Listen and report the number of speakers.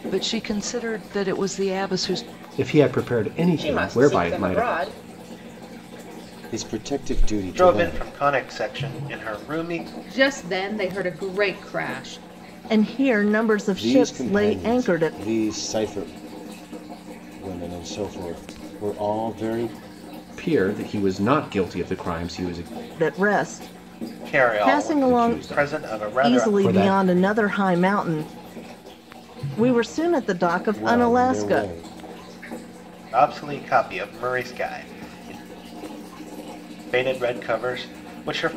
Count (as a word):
seven